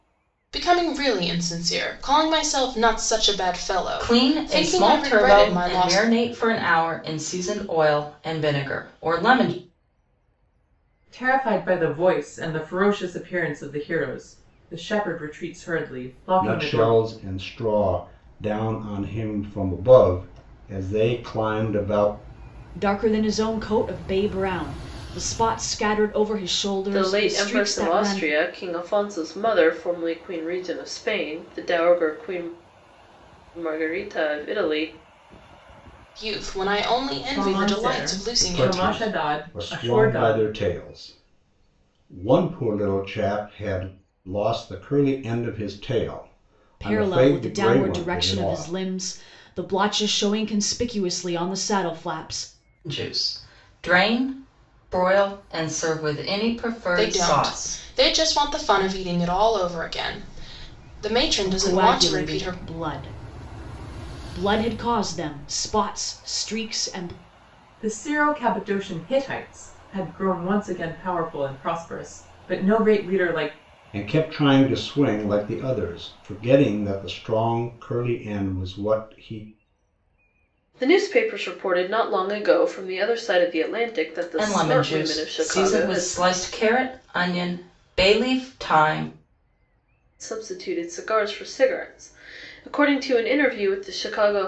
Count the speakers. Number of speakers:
six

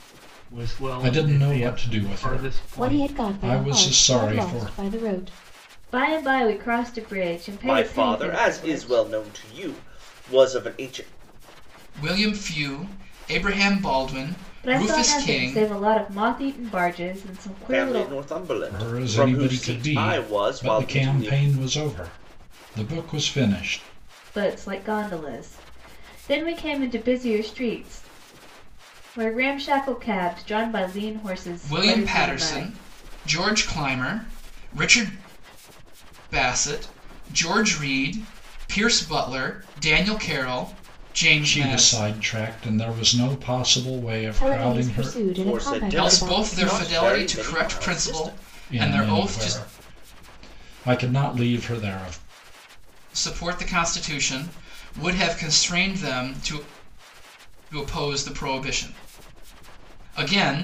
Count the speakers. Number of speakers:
six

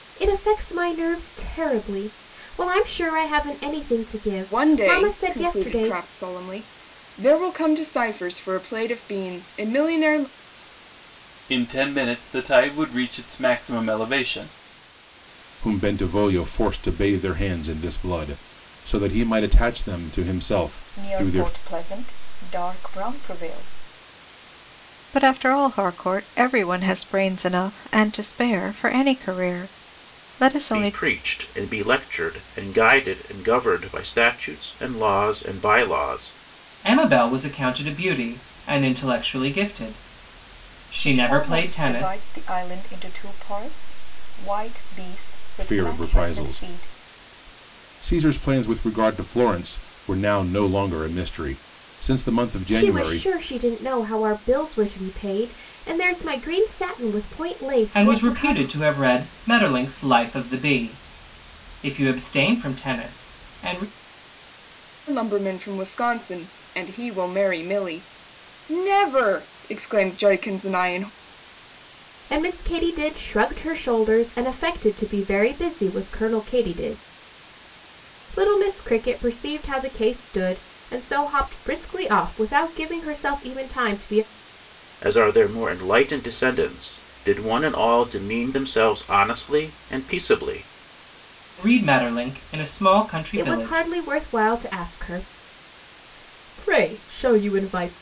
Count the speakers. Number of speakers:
eight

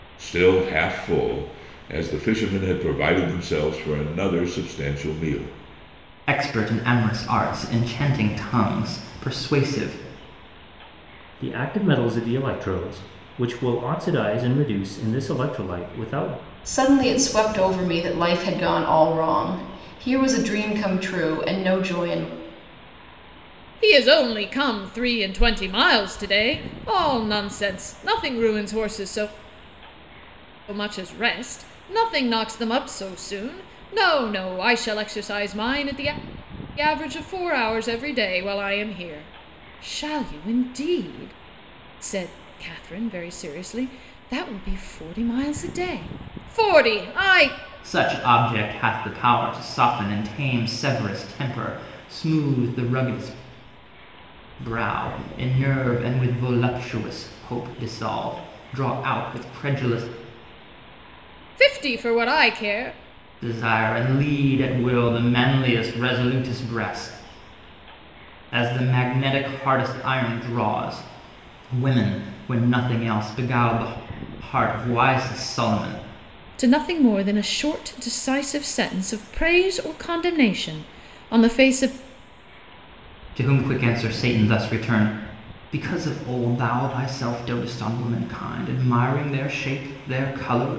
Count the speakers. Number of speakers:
five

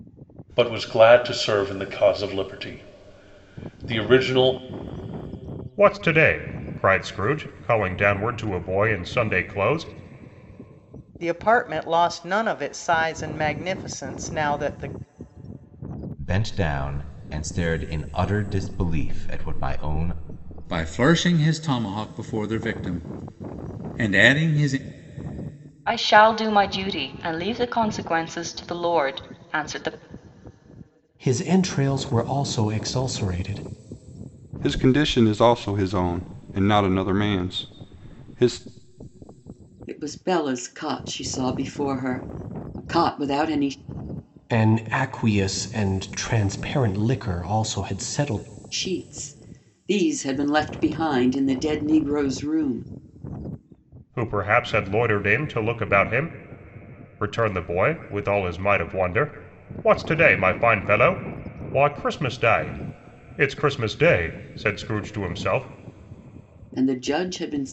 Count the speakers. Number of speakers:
nine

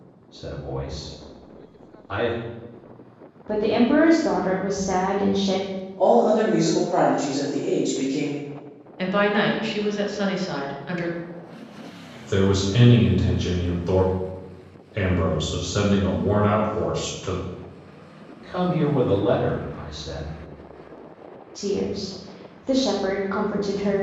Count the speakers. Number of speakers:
five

